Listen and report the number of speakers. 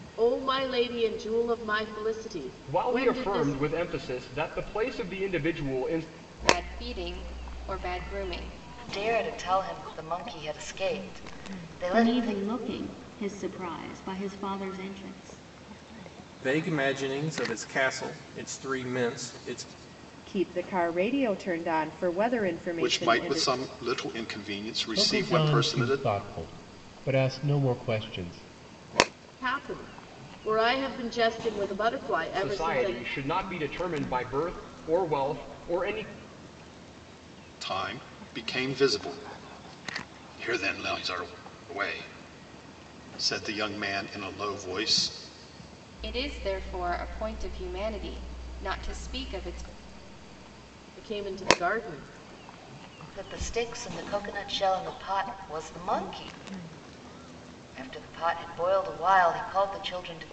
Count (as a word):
nine